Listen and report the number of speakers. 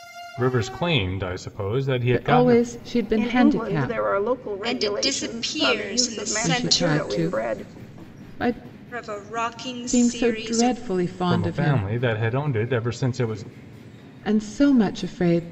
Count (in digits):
4